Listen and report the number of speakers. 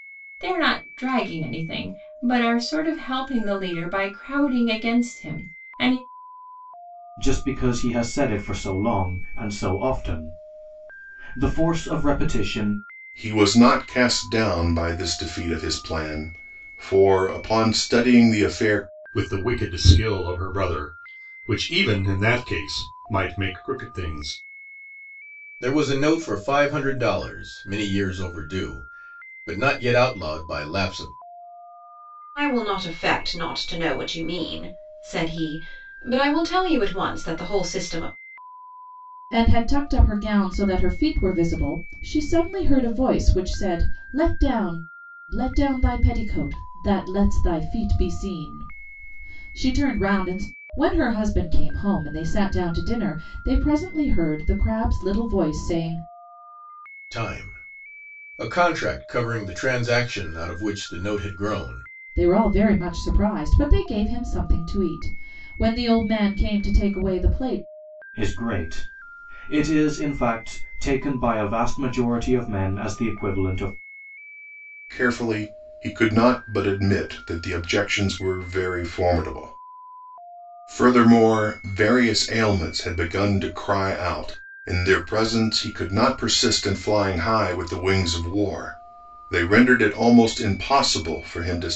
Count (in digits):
7